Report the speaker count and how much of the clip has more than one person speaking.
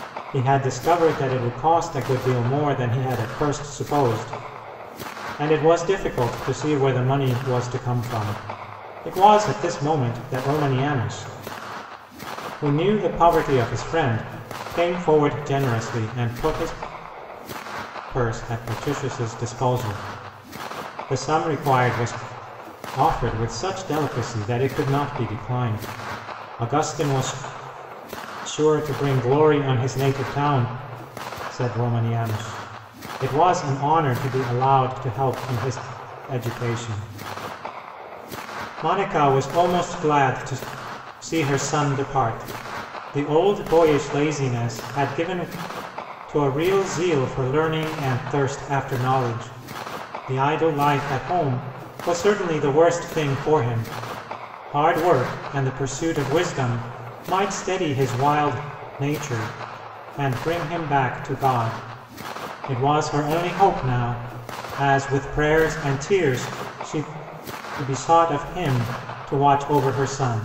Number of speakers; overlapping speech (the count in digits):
1, no overlap